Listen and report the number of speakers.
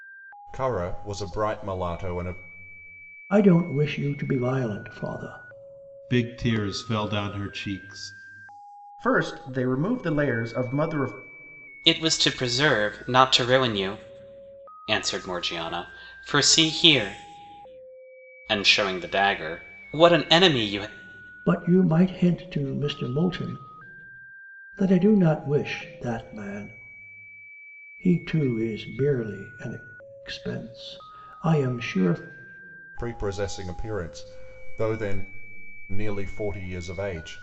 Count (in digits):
5